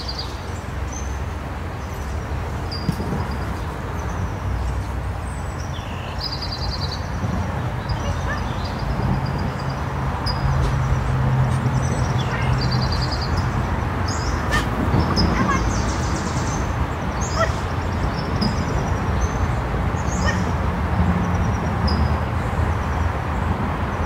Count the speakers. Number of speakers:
0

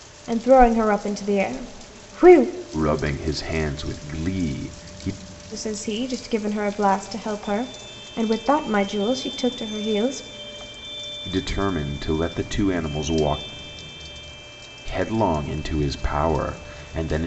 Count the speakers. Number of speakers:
2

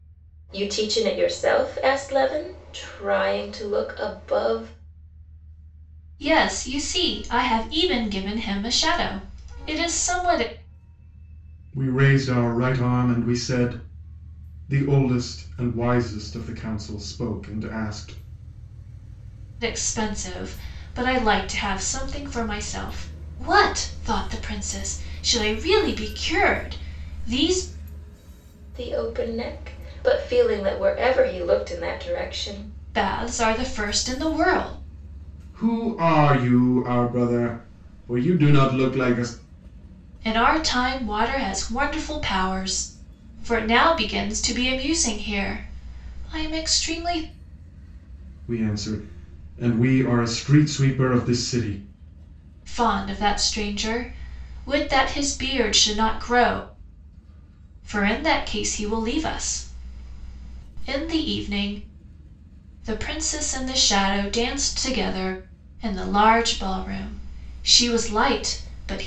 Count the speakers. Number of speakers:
3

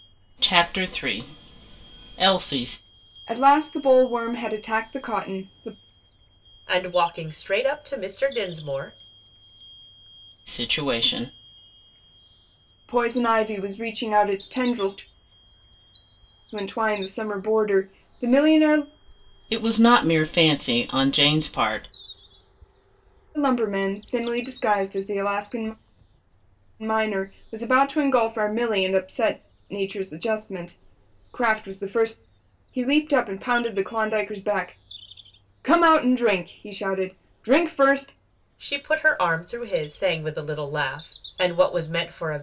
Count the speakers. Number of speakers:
3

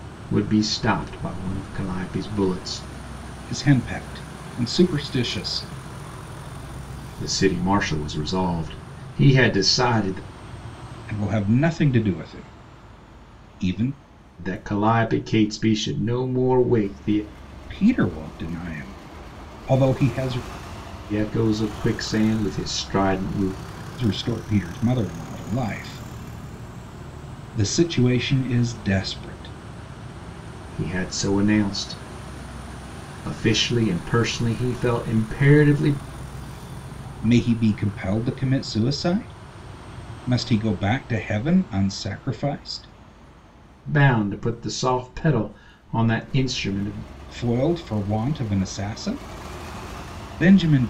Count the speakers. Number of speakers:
2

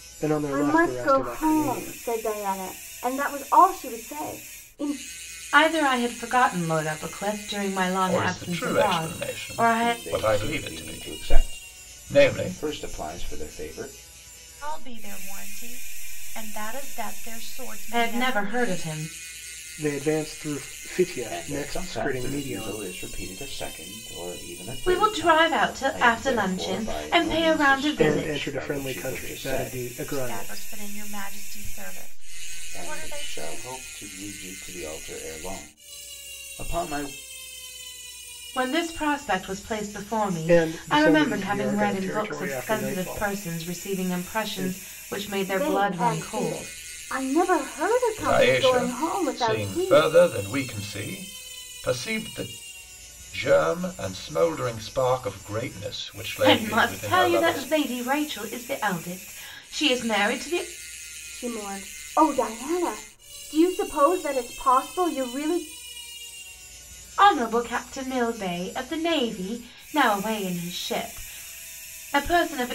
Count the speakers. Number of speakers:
6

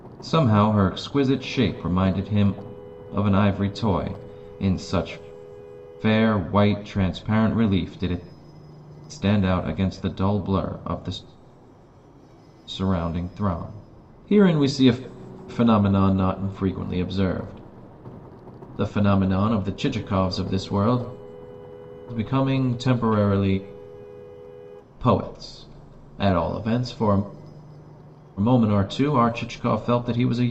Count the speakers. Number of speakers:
1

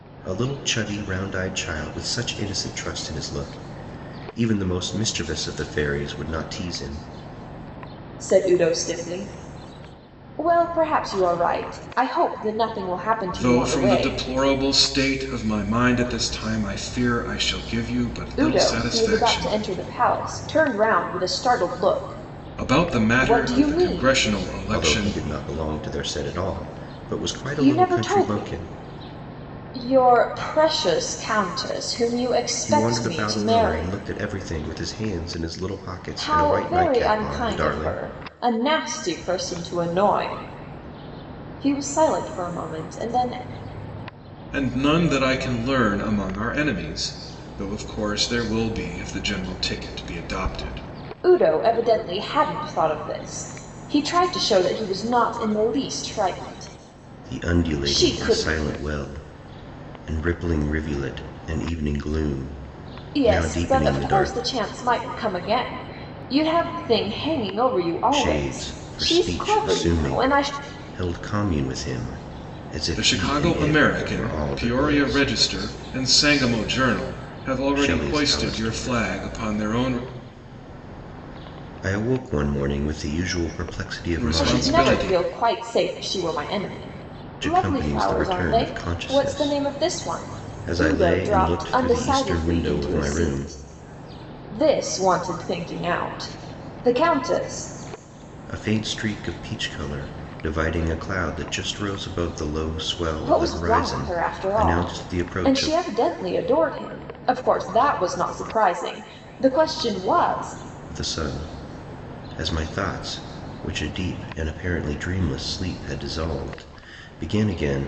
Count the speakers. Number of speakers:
3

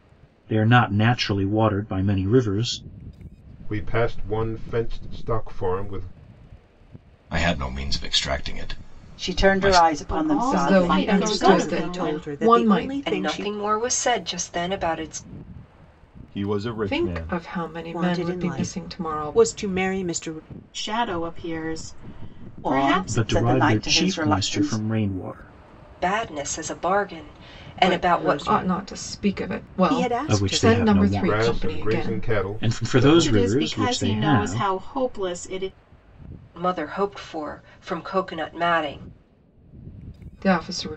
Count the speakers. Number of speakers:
9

